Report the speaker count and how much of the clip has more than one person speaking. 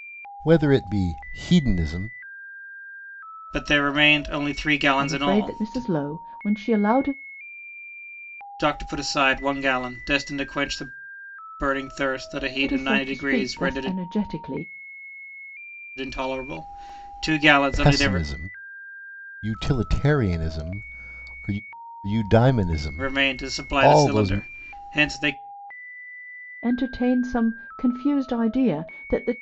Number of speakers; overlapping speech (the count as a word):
three, about 14%